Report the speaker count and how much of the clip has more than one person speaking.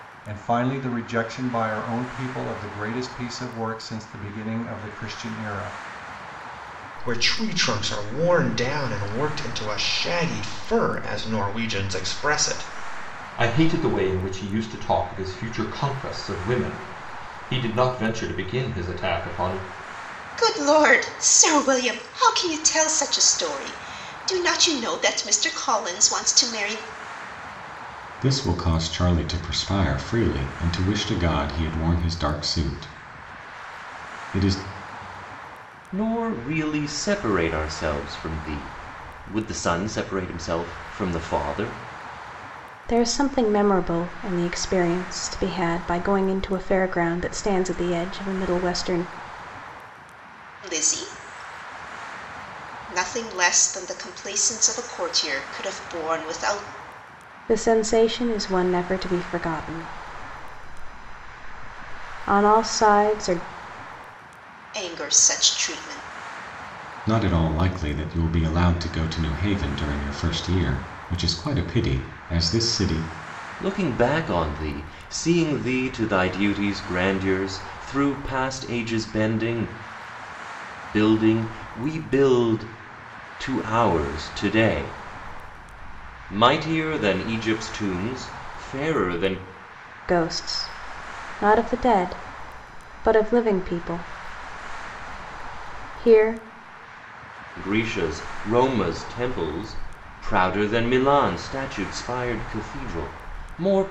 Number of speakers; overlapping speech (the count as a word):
seven, no overlap